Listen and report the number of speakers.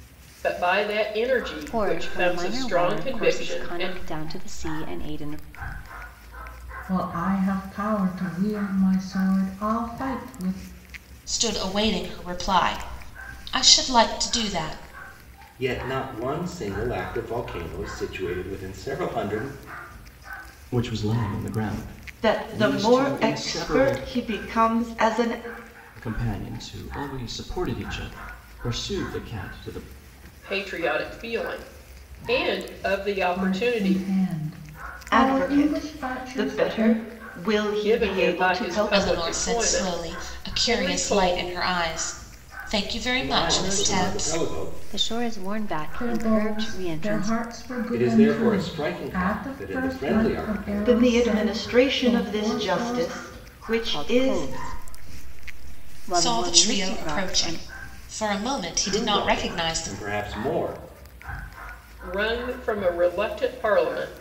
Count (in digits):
7